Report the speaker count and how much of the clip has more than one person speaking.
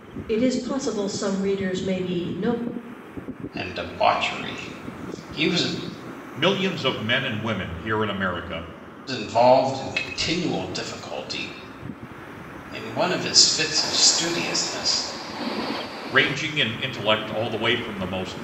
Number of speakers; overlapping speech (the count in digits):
3, no overlap